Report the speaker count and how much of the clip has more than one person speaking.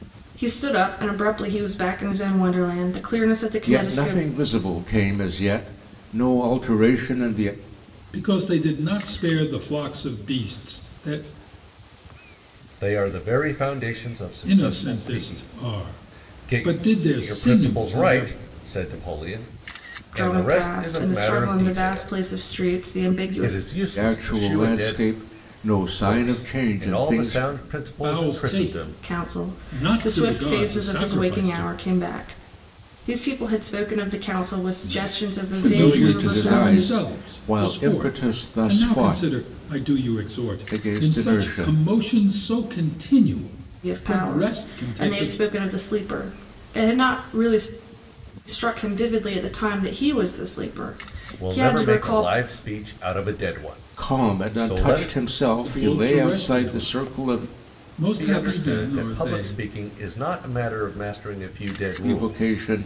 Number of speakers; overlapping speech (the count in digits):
4, about 43%